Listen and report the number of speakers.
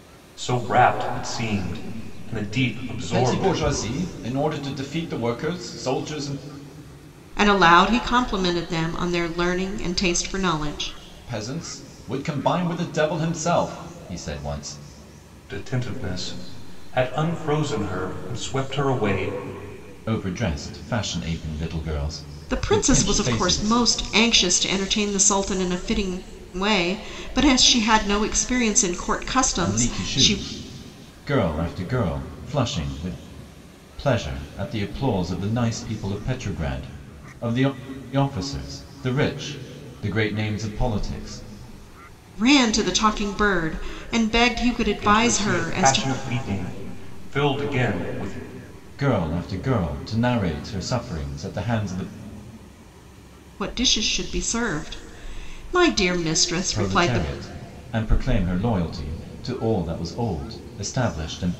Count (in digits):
3